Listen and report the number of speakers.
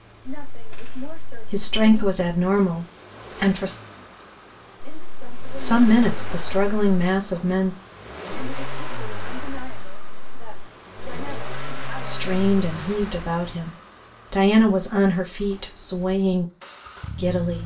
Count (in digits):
2